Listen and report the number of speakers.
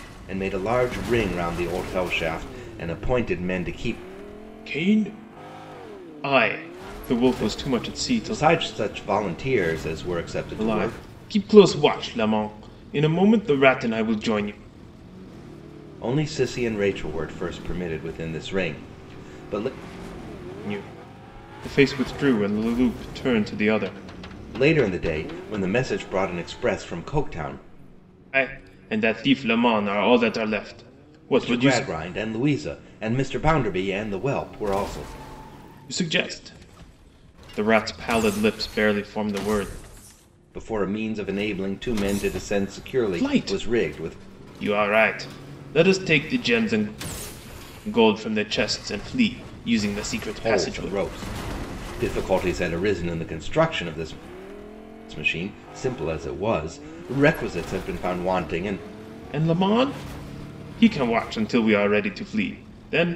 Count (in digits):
2